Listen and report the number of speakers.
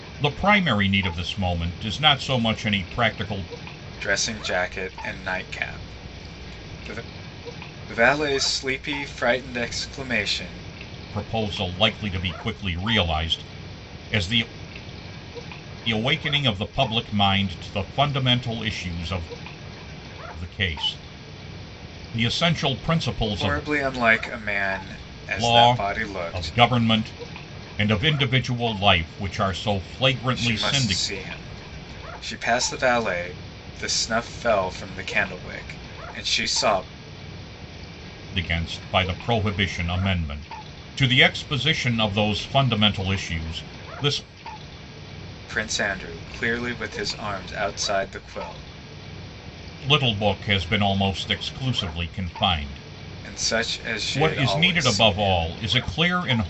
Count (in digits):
2